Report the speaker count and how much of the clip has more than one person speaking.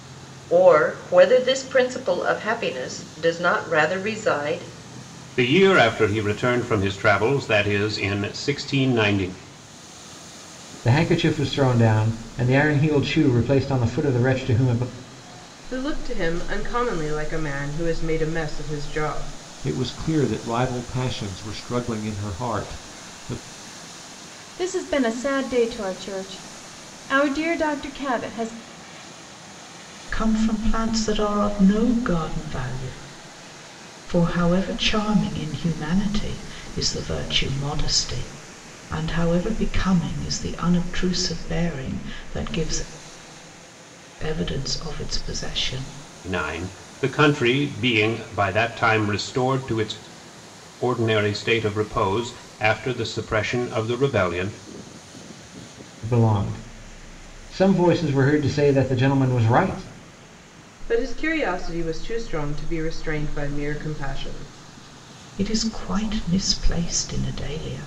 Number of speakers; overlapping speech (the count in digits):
7, no overlap